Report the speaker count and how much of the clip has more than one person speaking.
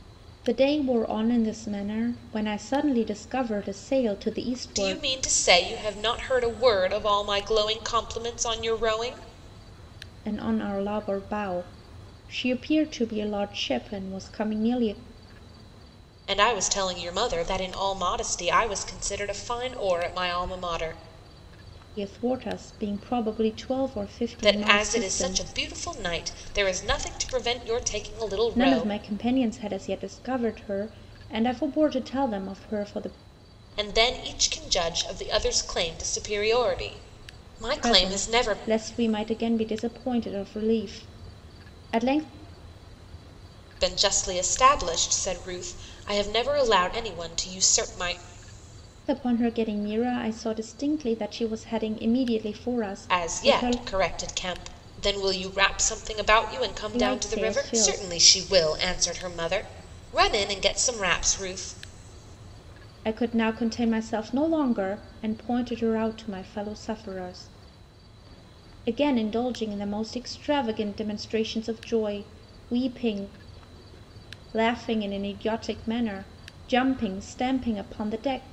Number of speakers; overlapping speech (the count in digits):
2, about 6%